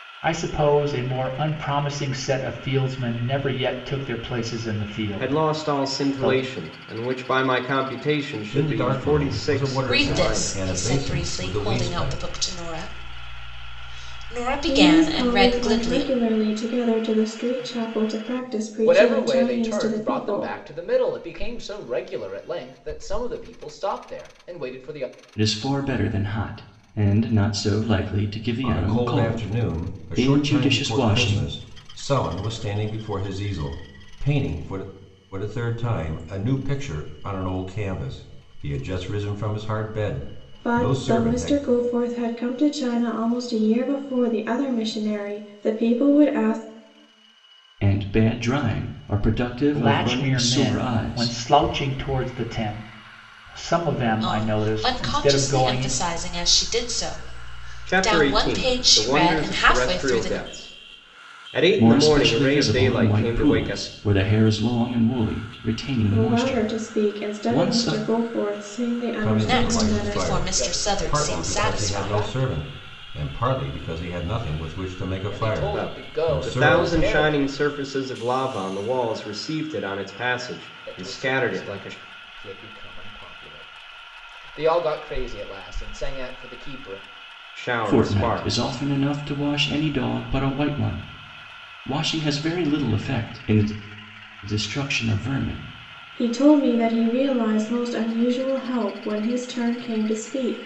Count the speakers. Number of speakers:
7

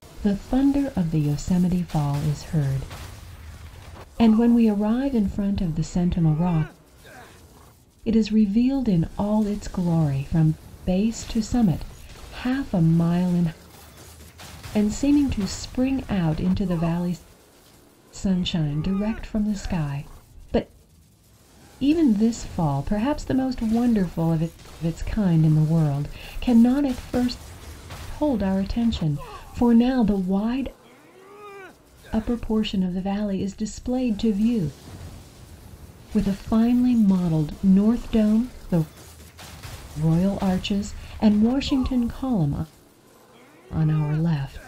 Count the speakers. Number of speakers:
1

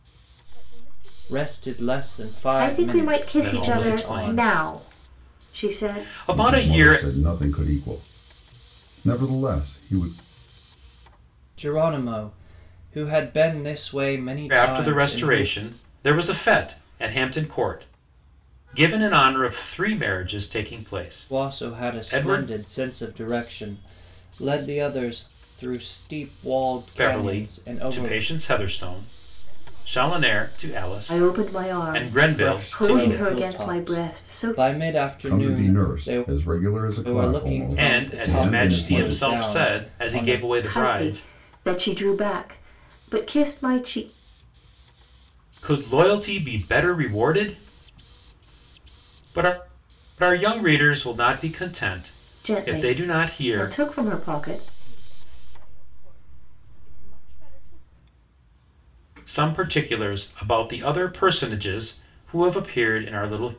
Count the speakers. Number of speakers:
5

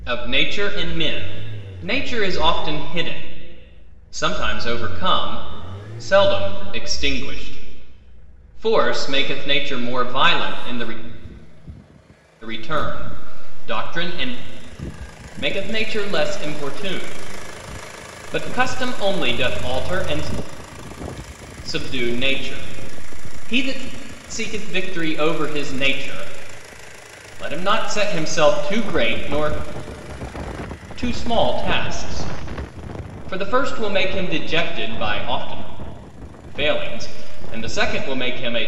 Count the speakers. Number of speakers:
1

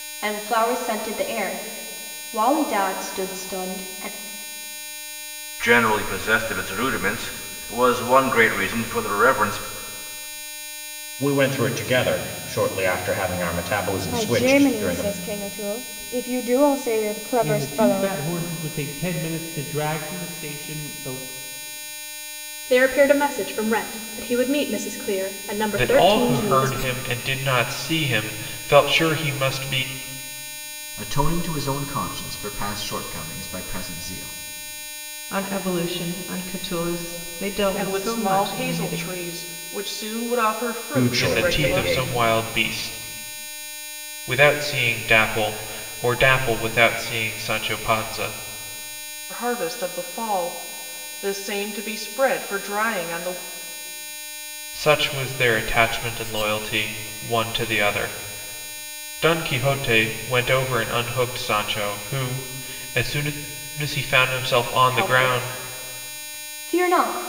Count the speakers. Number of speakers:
10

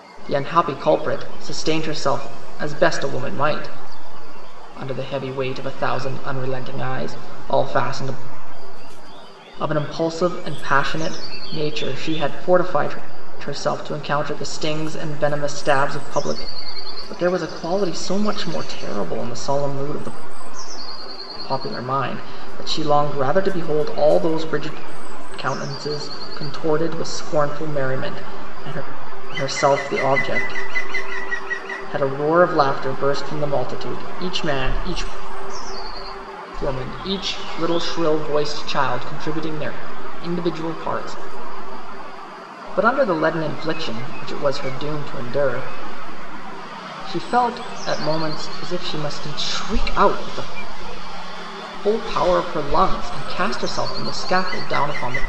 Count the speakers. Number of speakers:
1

